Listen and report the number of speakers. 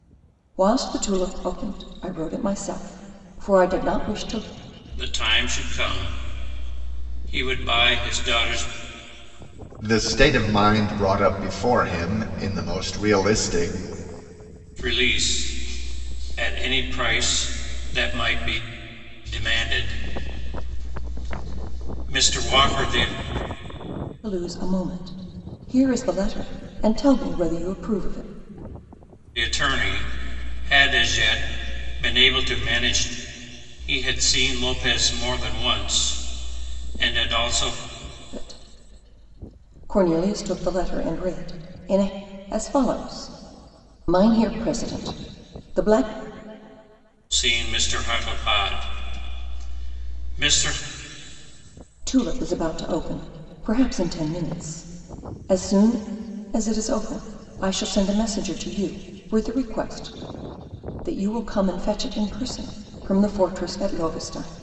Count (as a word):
three